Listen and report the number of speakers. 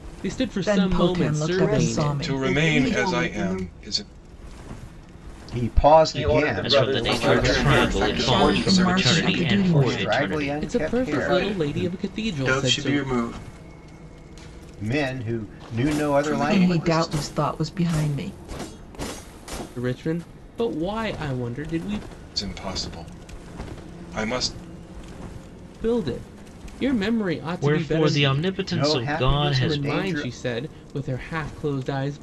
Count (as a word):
eight